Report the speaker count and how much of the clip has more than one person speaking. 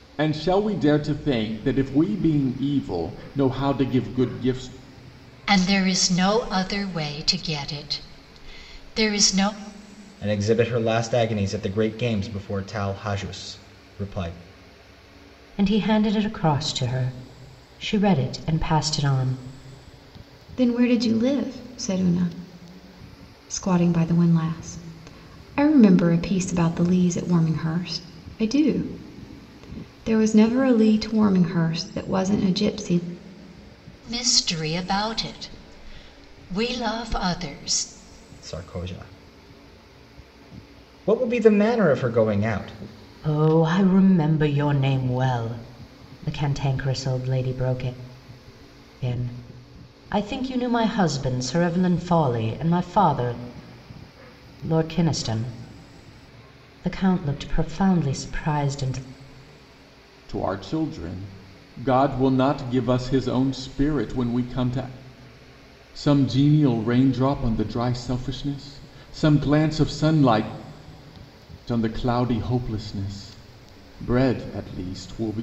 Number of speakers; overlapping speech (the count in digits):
5, no overlap